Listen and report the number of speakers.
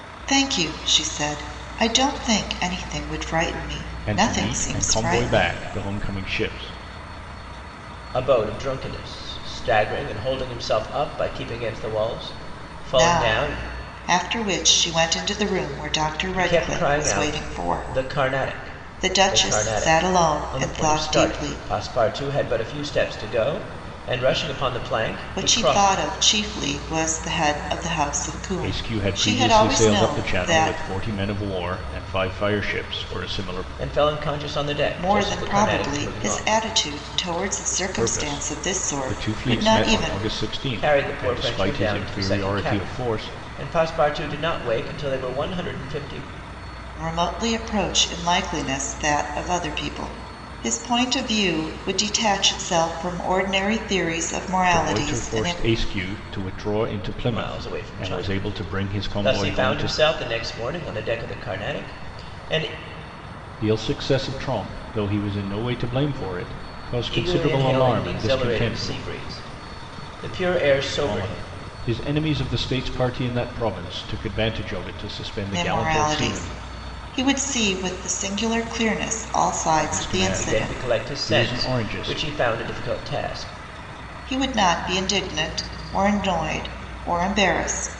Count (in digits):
3